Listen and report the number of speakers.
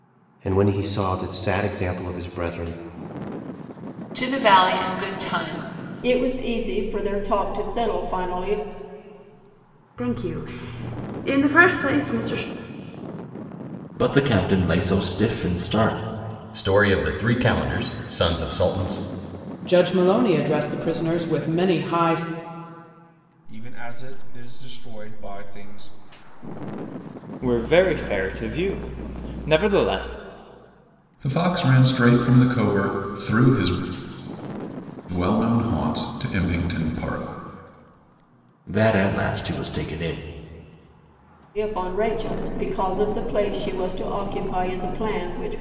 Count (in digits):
10